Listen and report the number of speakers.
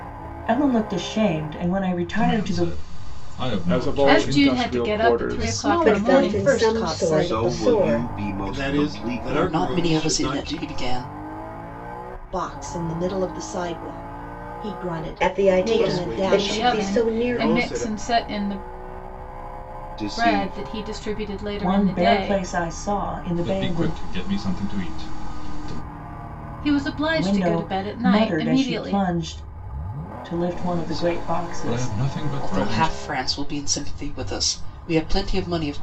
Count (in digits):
9